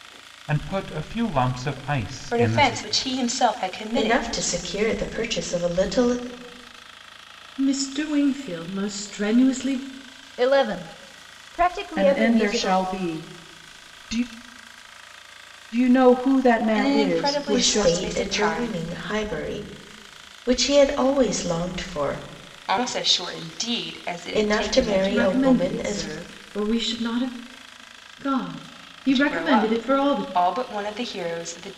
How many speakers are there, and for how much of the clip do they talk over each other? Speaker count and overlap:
6, about 22%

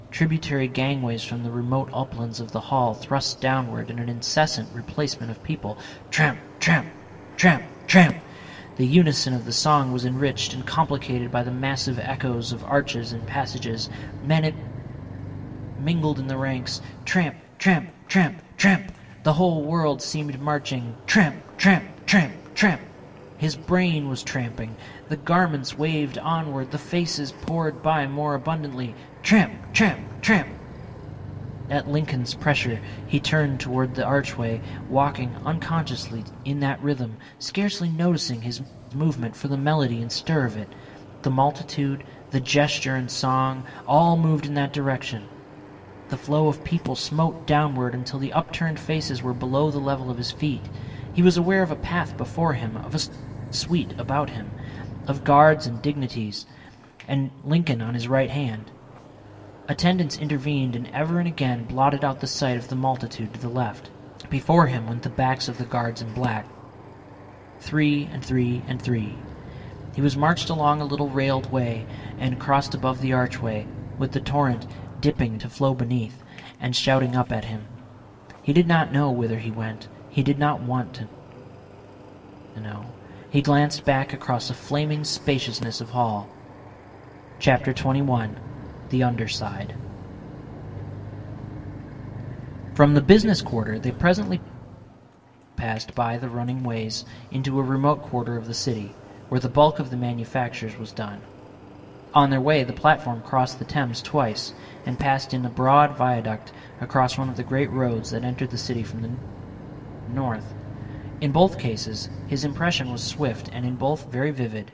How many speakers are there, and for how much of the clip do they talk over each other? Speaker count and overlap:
1, no overlap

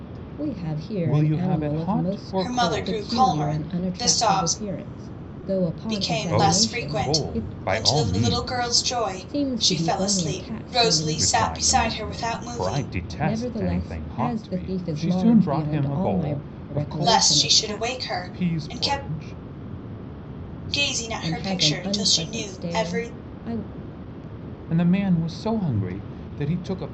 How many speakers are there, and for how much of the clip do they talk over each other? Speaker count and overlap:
3, about 66%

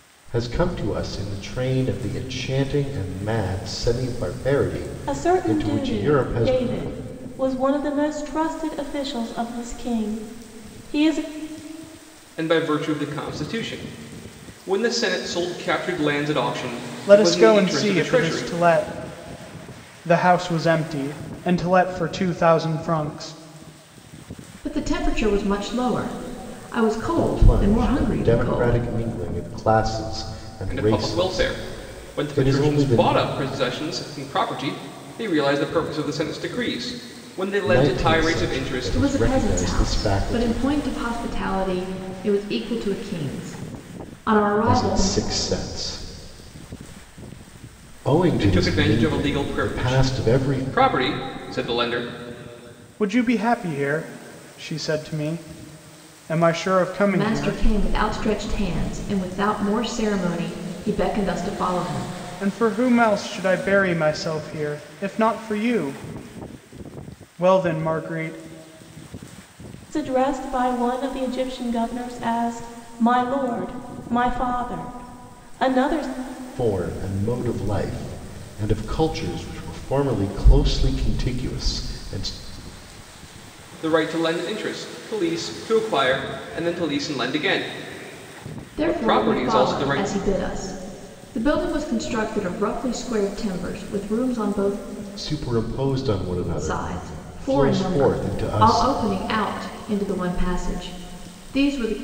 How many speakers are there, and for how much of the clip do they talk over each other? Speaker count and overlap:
5, about 17%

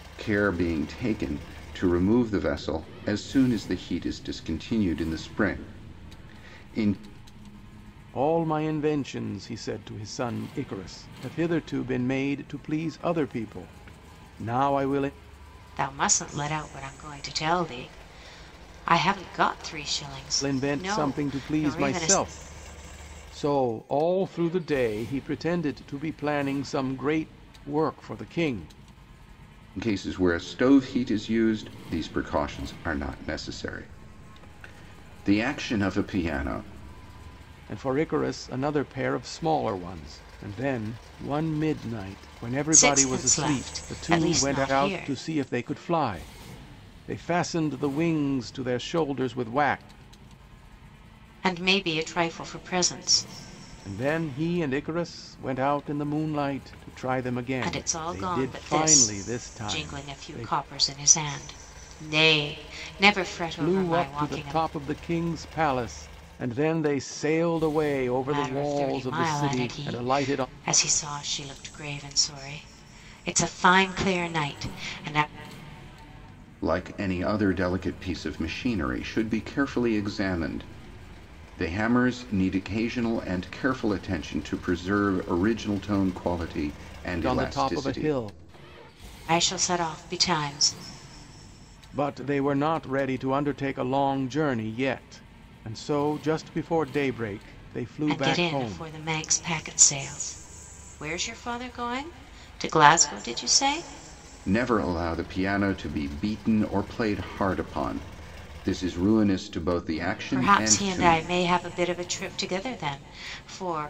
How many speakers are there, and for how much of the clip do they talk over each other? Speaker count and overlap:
3, about 12%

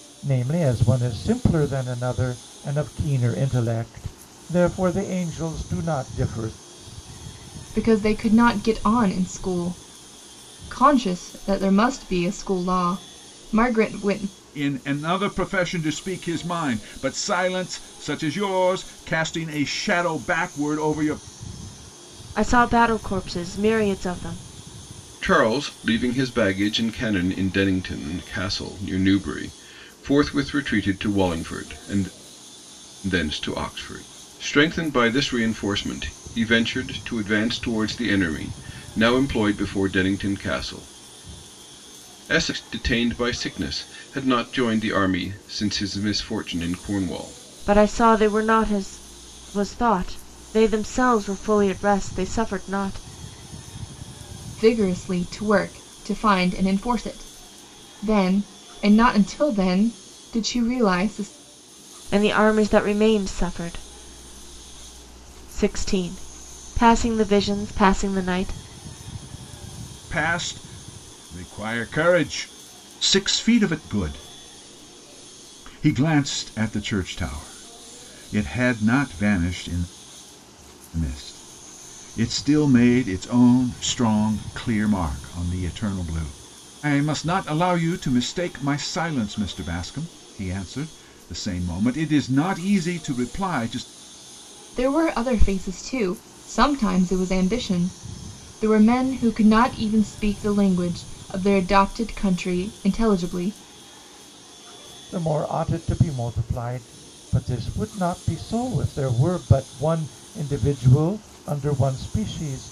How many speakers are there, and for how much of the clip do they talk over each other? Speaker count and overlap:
5, no overlap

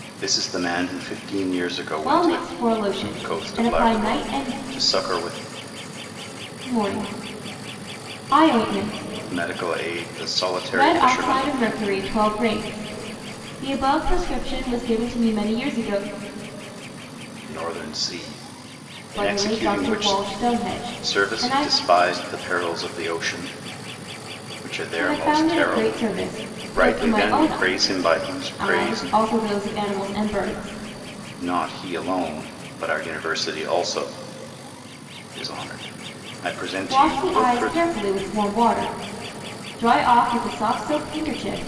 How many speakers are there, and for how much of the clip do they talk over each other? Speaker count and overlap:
2, about 20%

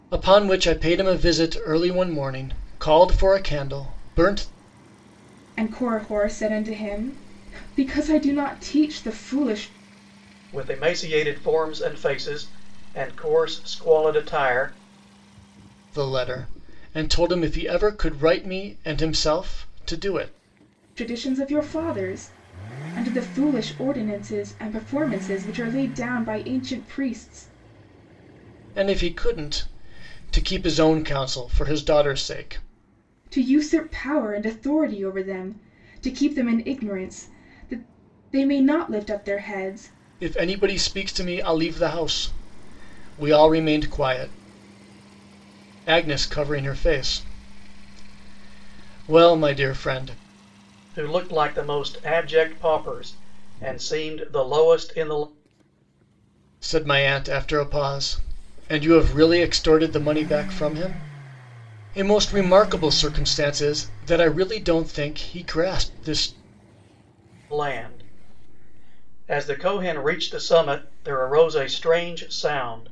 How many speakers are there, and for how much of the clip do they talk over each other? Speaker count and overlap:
3, no overlap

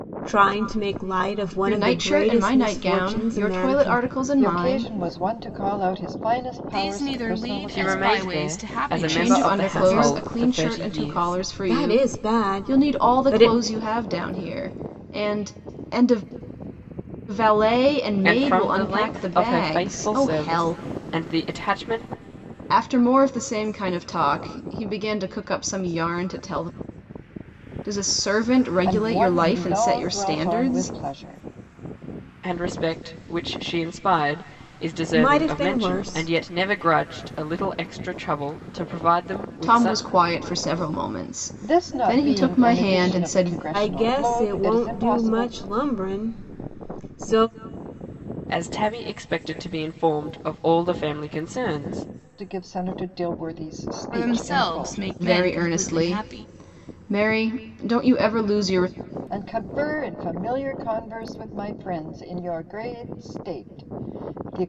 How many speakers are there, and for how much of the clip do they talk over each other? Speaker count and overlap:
5, about 34%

